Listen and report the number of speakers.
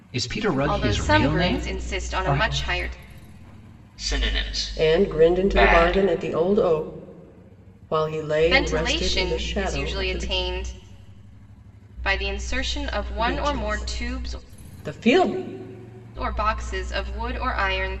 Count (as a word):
four